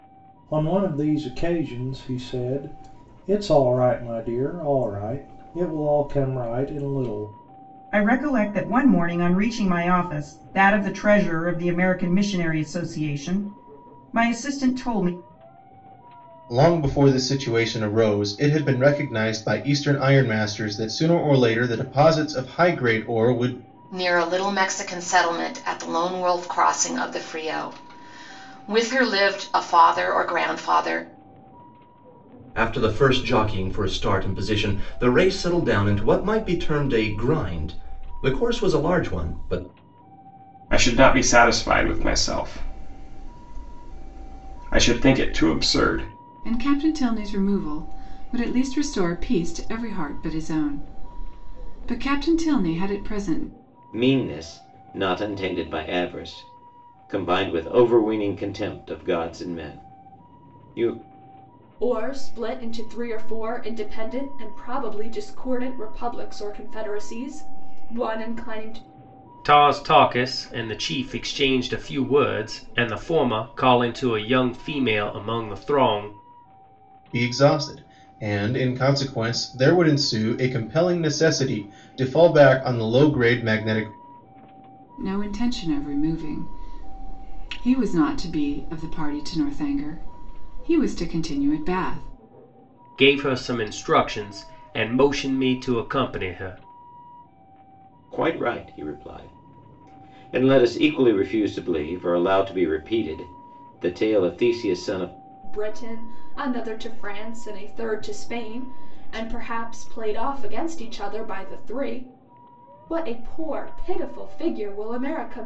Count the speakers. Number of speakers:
ten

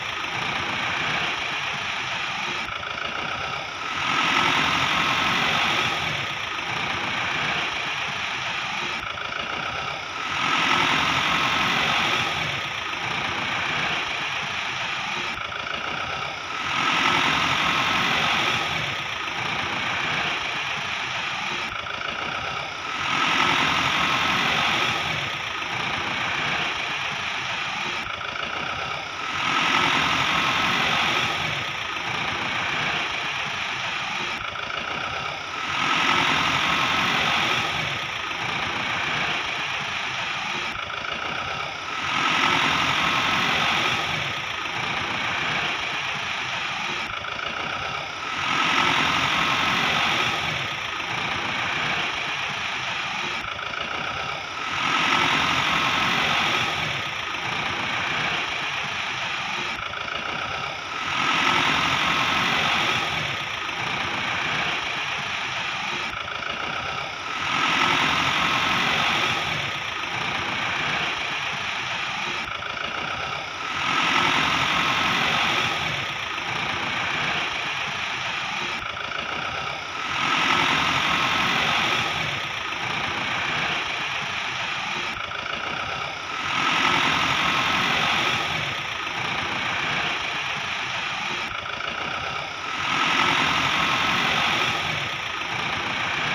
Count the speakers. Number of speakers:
zero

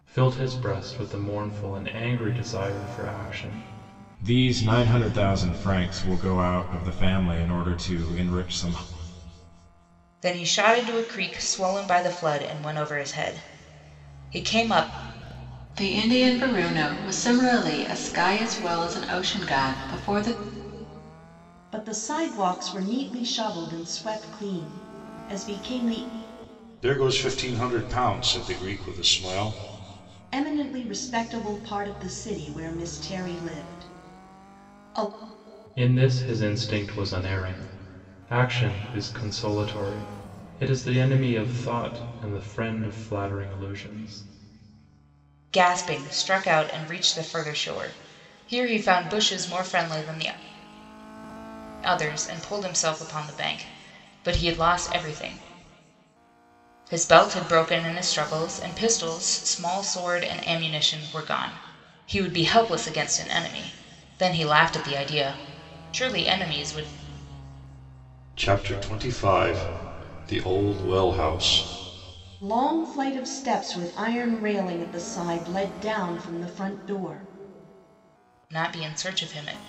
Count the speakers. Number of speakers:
six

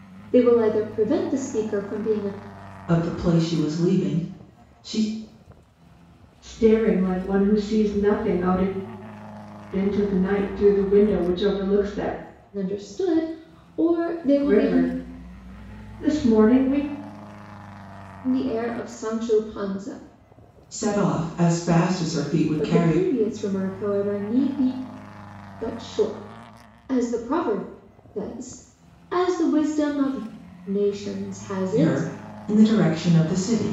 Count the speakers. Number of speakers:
three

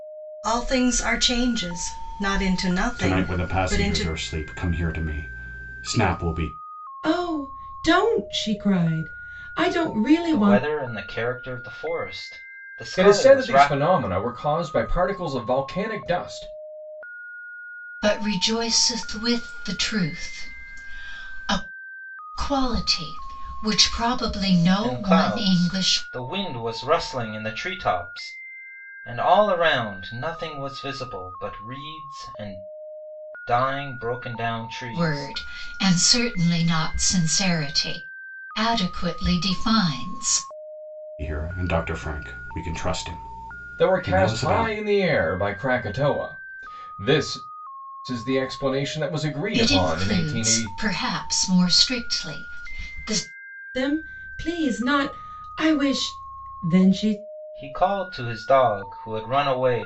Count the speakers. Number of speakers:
six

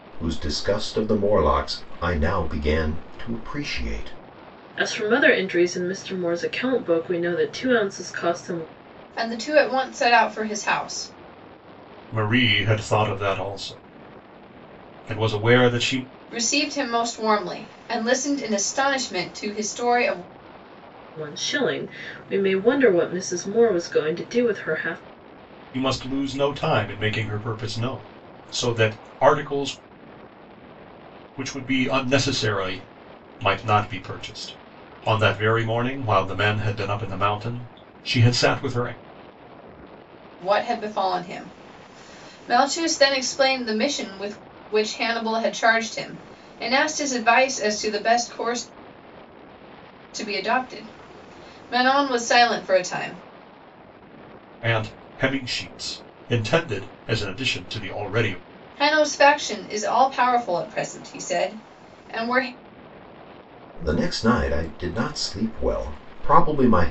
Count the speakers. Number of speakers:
four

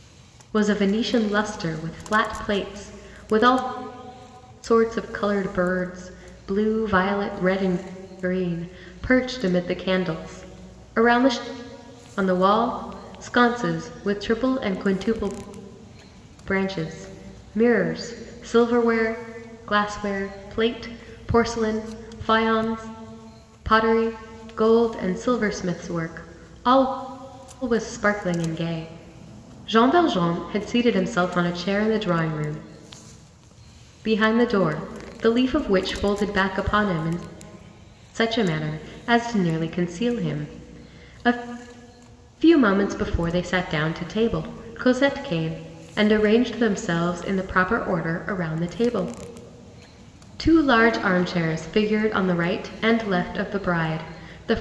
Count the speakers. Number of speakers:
one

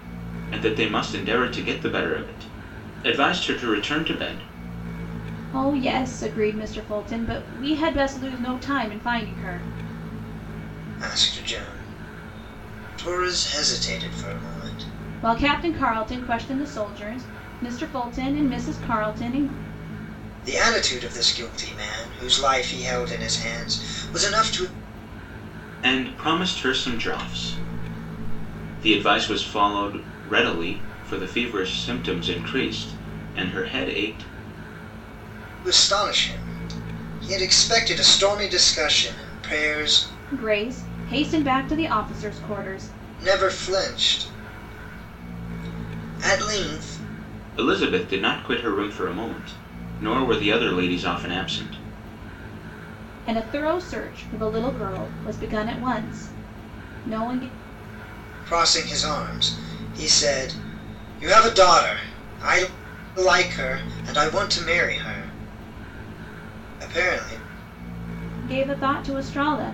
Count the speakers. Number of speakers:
three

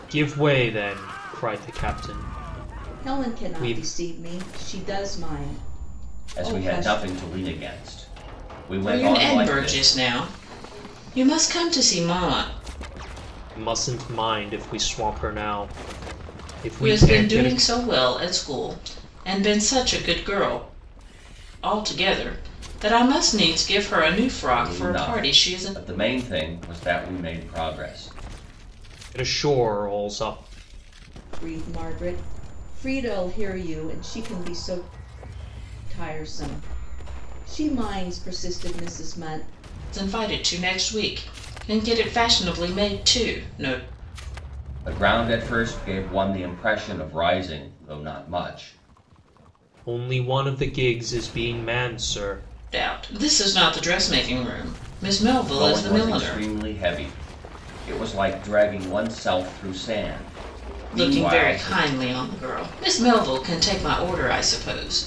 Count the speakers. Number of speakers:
four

